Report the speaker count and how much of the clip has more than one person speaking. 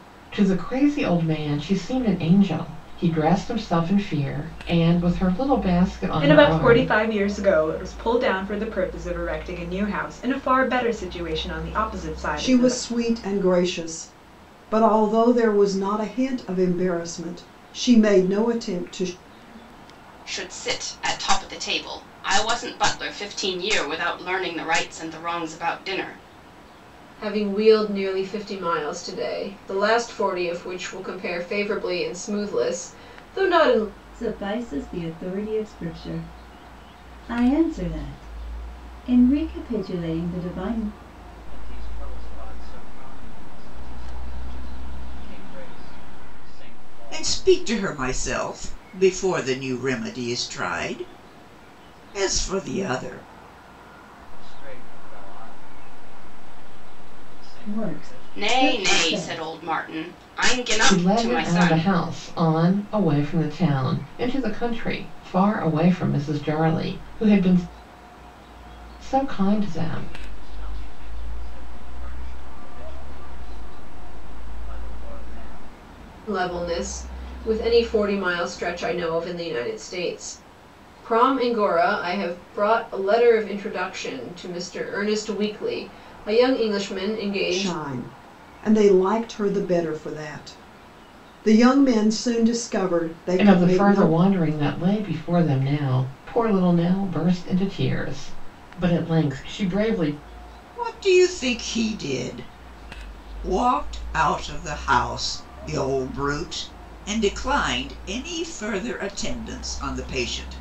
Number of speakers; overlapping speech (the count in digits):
8, about 6%